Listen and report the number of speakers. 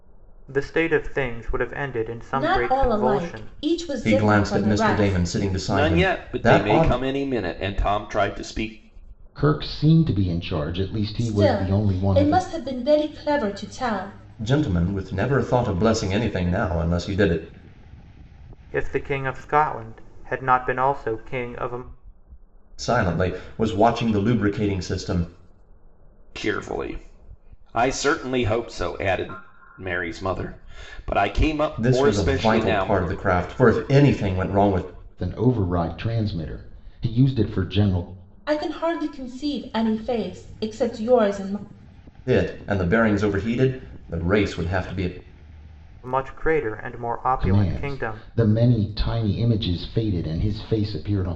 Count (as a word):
five